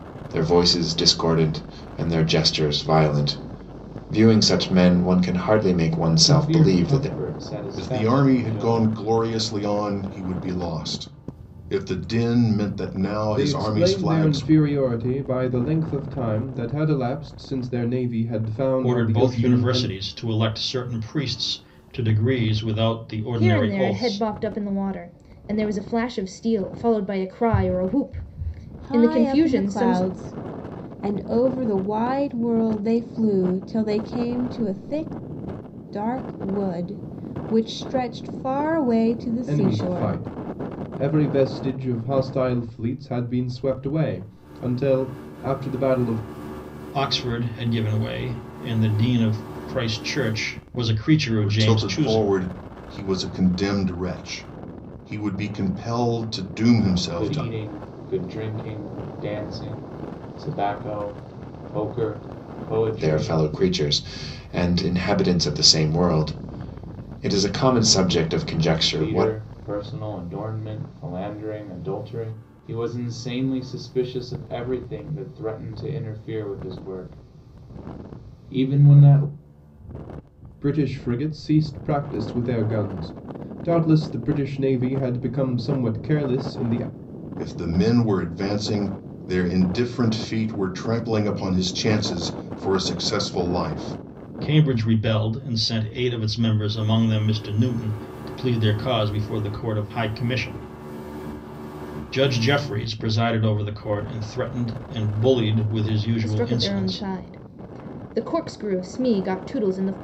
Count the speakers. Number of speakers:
7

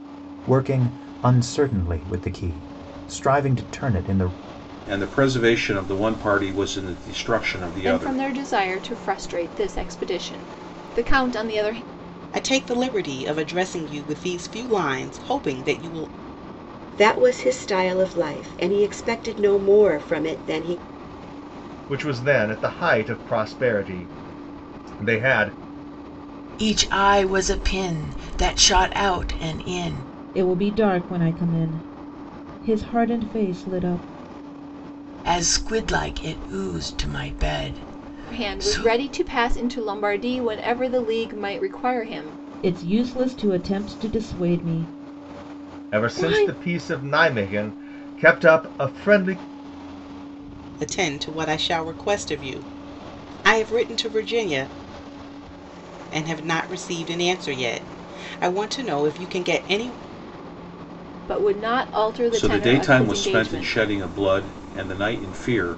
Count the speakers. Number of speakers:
8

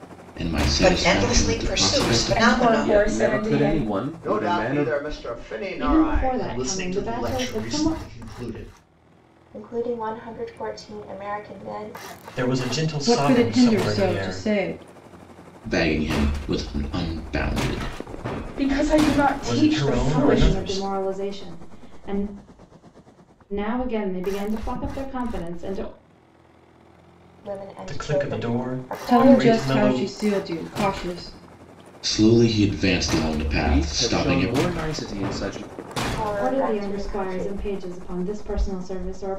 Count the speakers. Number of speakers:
10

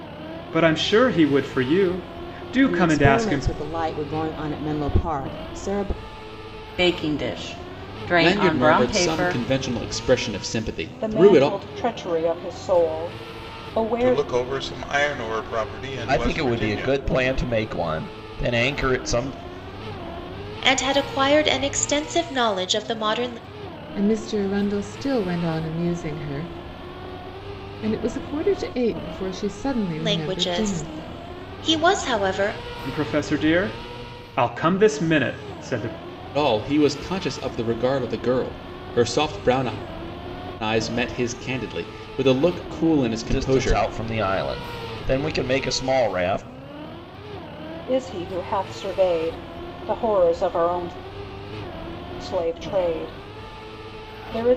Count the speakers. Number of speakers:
9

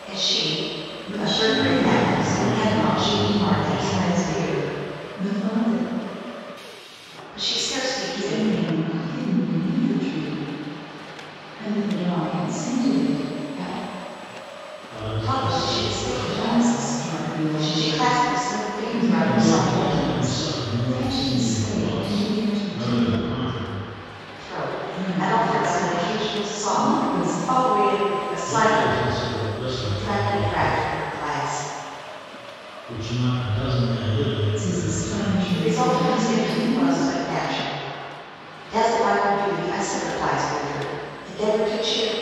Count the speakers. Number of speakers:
3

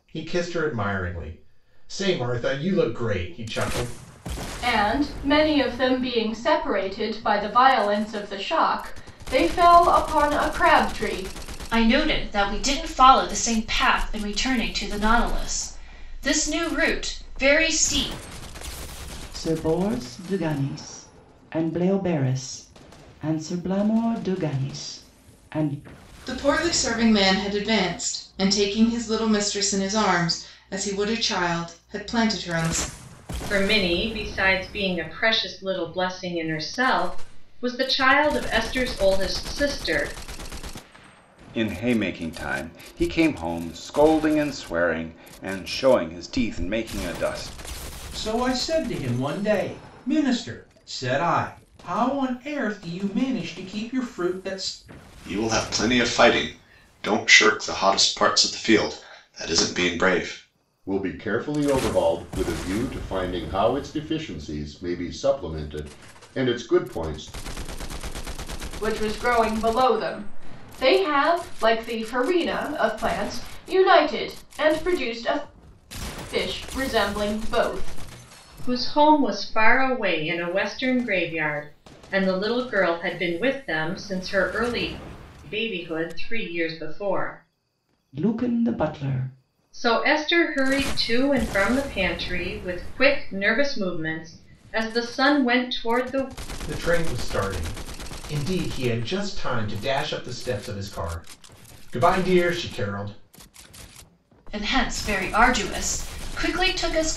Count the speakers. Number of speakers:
10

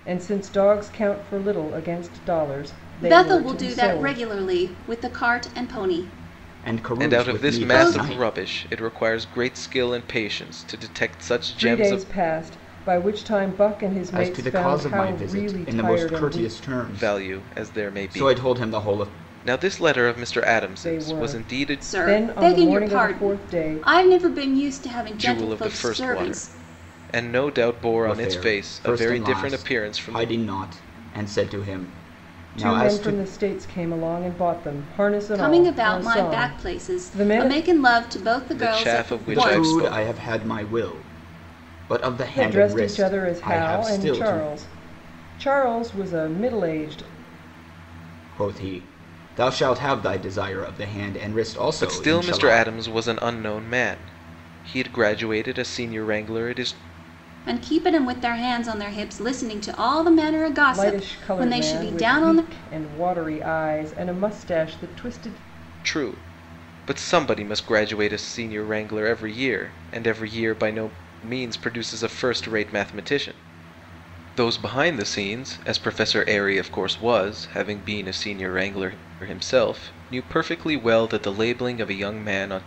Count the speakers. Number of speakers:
4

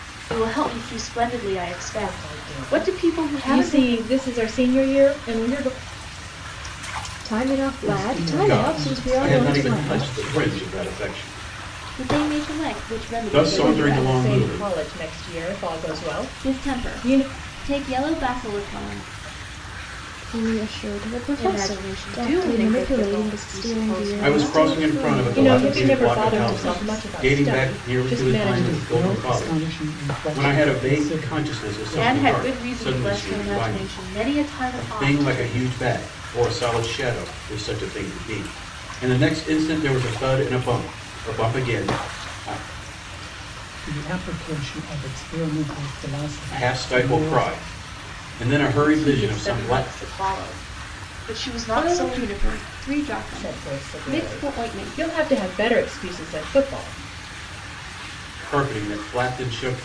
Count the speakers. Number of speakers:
6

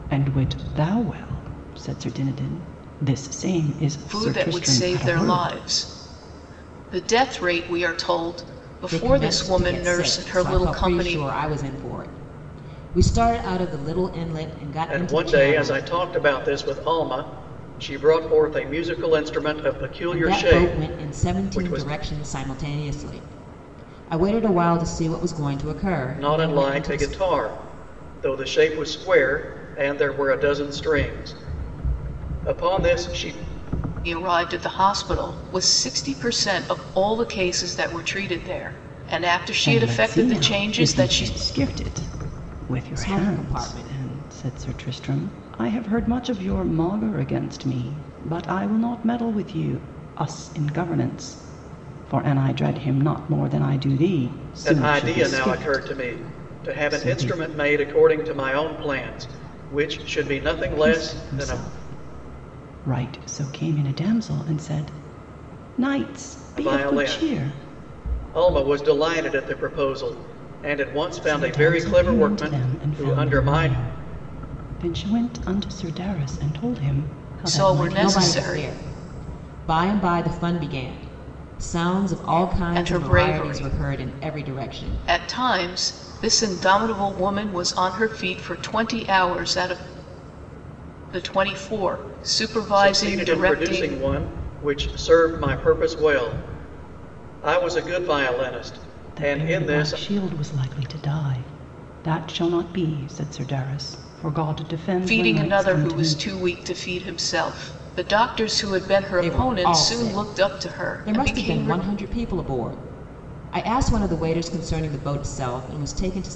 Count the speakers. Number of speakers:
4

